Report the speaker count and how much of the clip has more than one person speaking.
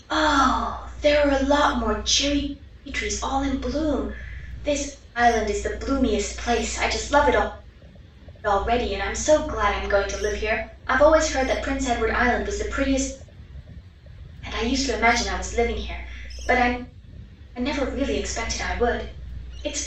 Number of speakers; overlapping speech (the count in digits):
1, no overlap